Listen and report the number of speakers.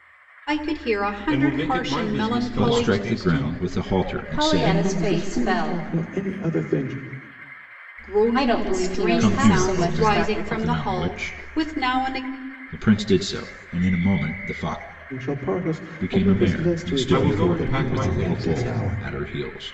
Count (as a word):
five